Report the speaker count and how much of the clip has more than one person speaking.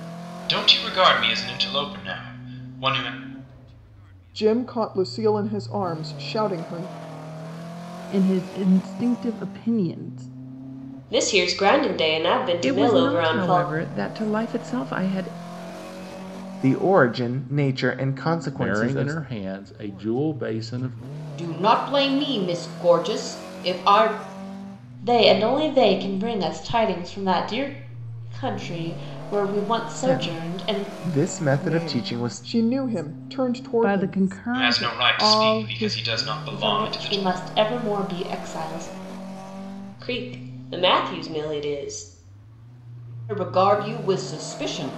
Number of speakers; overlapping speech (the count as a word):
nine, about 14%